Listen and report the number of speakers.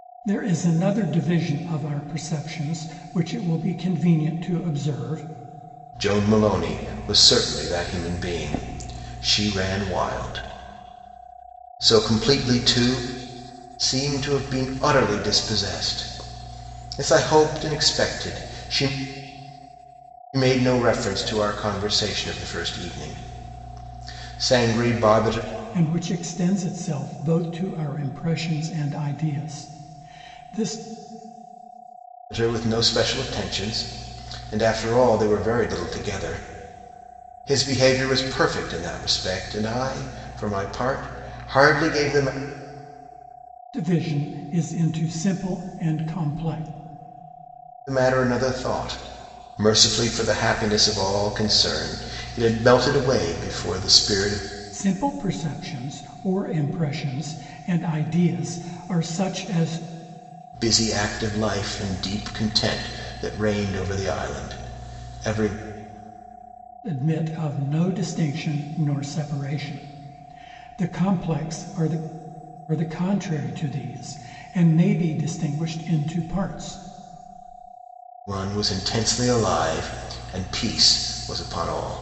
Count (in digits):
2